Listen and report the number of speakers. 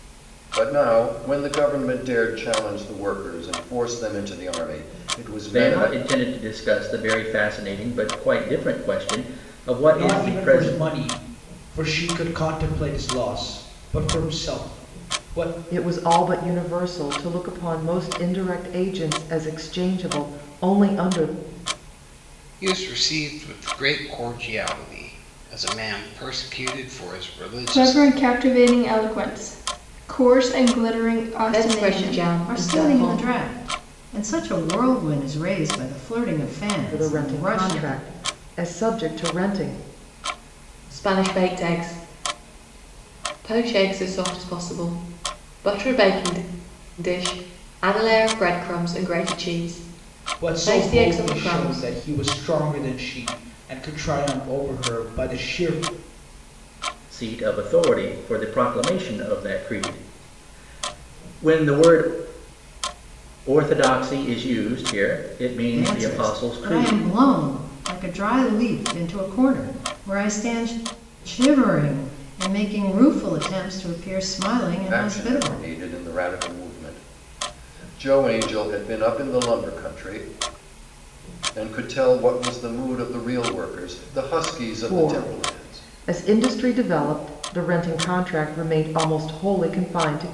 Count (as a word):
eight